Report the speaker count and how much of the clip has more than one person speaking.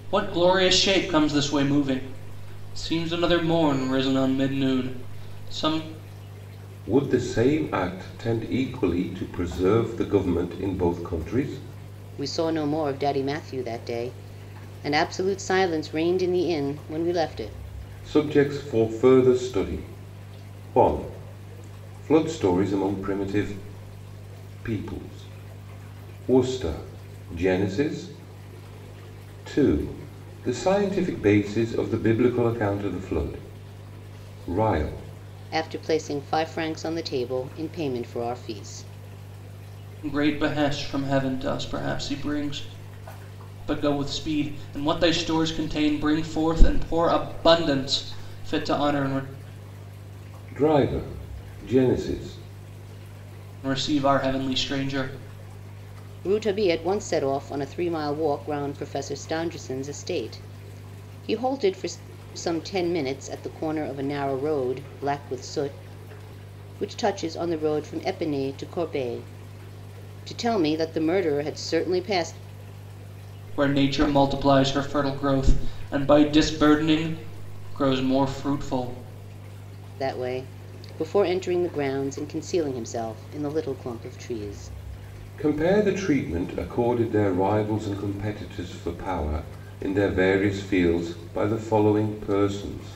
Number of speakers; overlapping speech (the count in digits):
3, no overlap